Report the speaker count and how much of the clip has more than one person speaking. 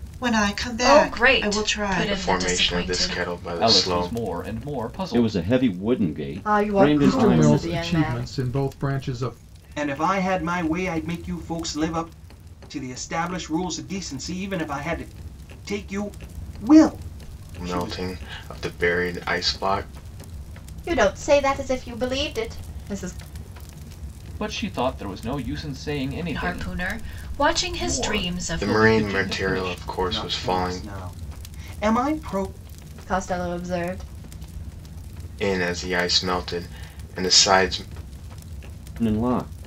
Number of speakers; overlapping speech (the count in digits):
8, about 22%